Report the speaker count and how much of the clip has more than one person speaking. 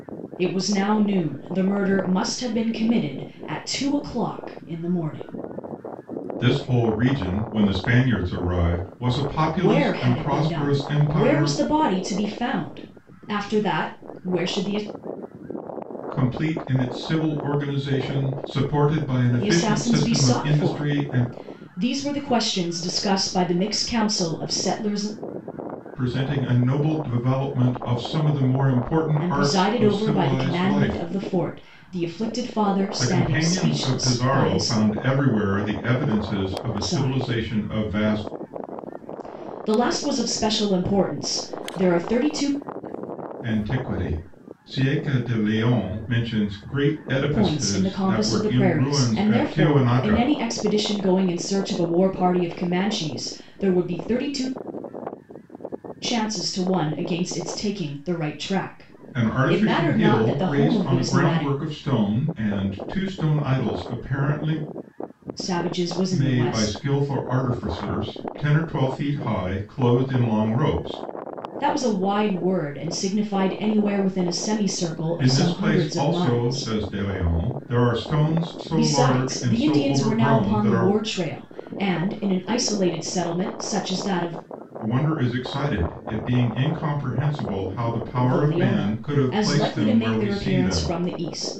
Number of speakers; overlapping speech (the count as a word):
two, about 24%